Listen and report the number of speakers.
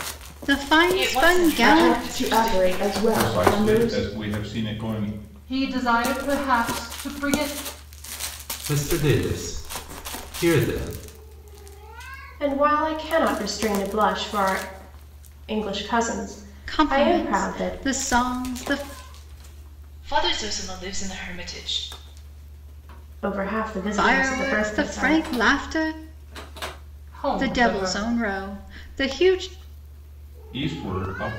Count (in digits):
7